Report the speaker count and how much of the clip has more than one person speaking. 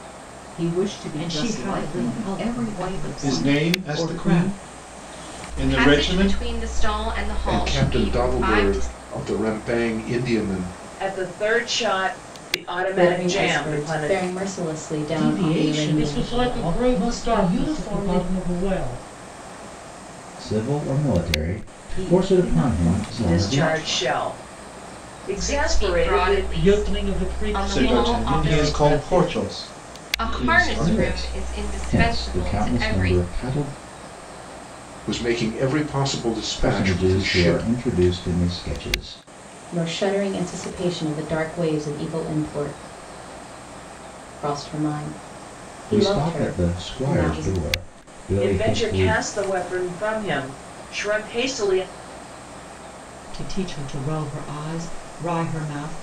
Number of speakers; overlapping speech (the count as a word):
ten, about 42%